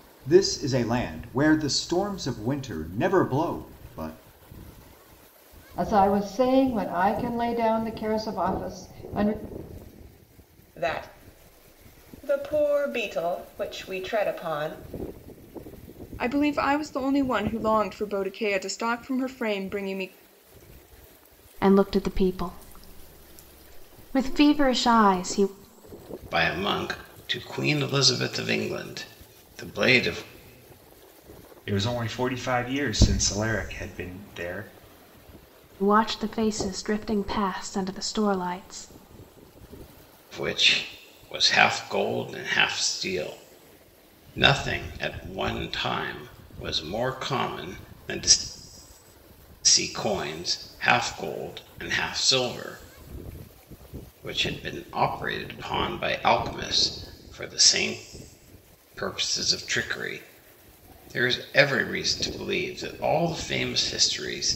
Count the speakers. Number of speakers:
7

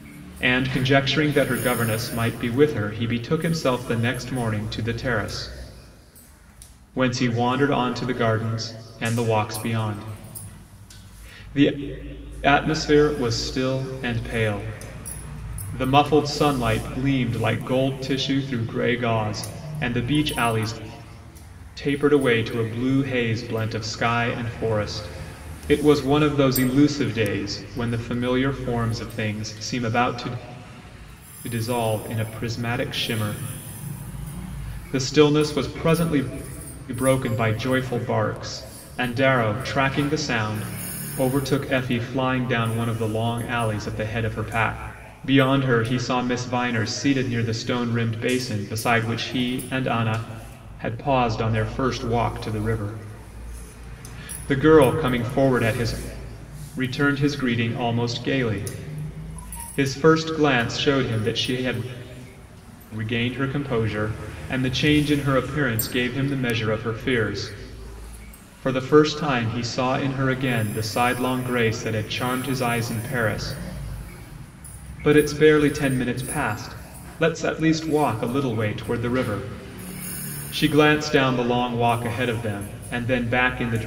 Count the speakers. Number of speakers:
1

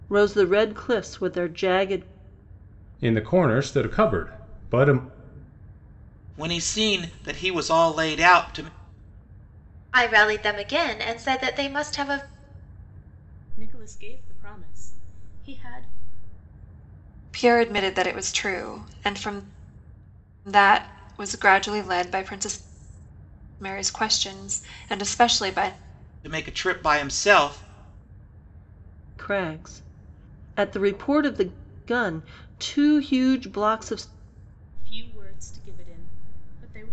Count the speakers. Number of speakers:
6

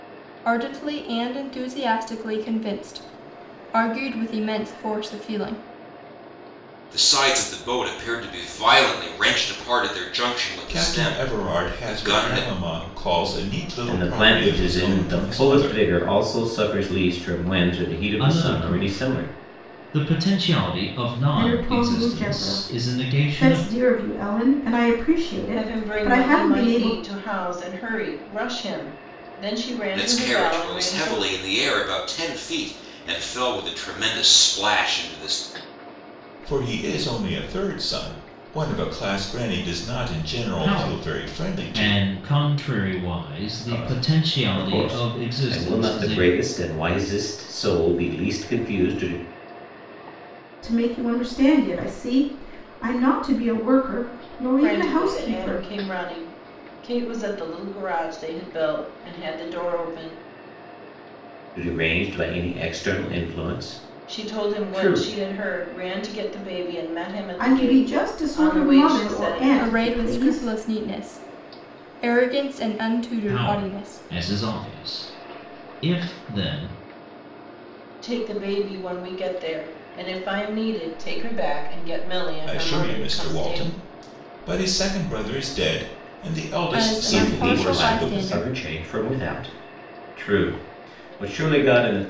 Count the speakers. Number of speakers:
7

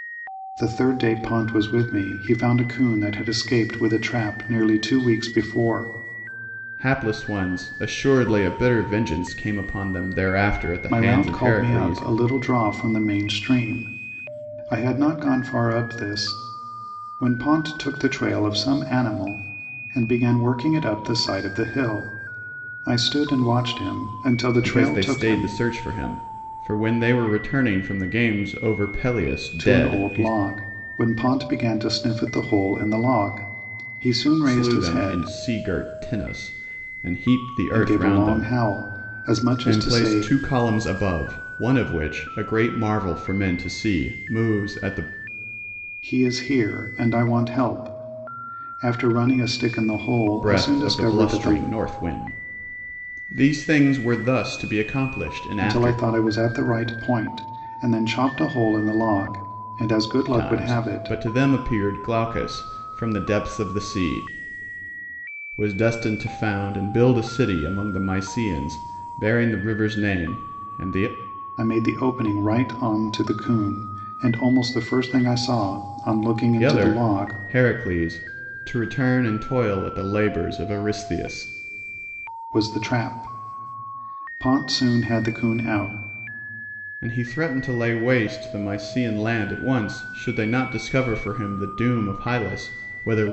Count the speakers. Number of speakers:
2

